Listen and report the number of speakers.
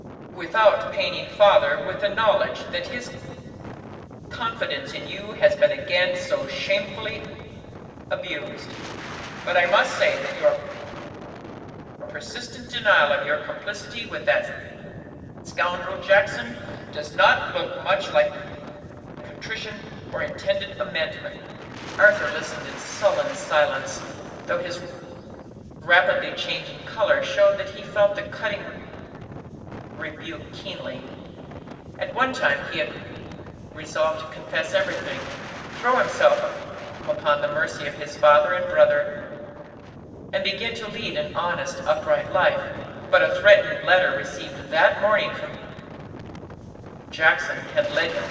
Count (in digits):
1